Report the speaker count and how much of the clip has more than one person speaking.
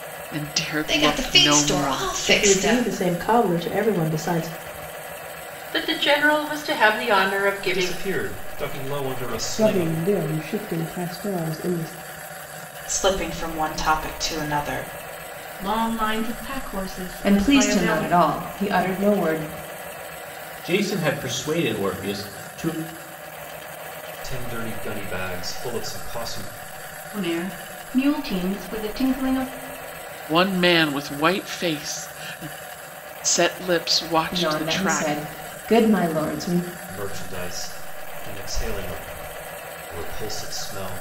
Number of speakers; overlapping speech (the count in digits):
10, about 12%